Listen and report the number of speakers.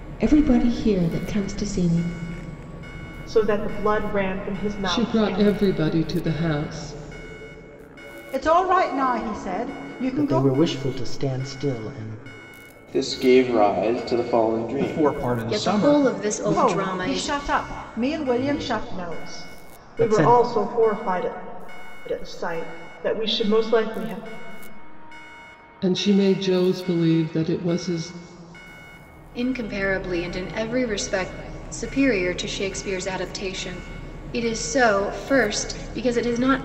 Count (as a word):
eight